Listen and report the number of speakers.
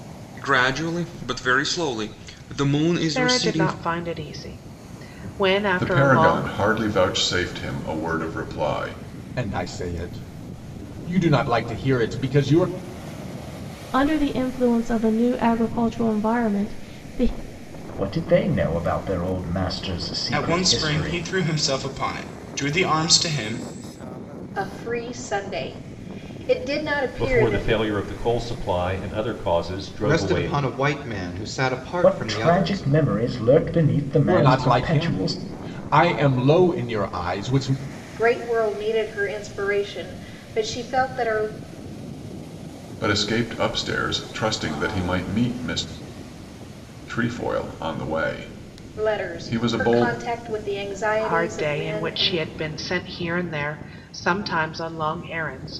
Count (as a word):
ten